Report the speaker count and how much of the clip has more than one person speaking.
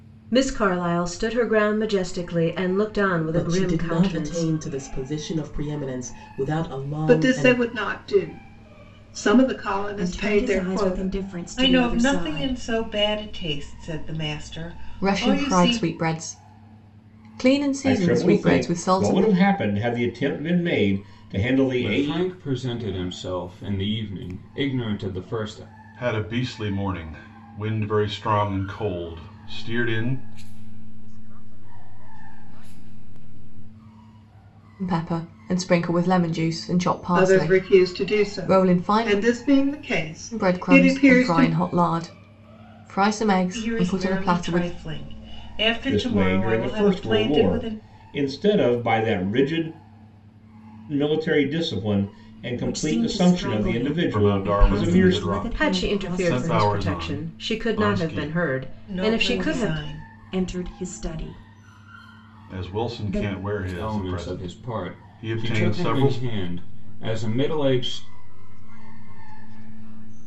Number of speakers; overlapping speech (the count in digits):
10, about 37%